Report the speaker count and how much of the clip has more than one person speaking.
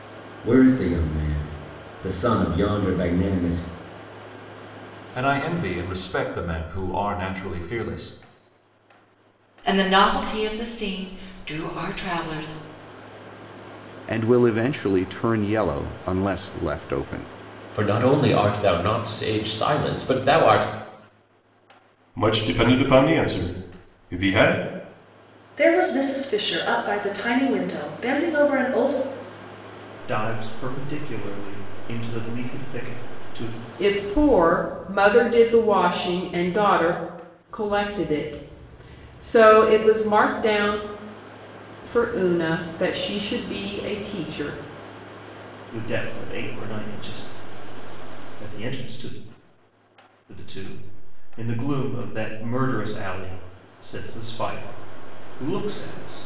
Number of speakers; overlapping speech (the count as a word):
nine, no overlap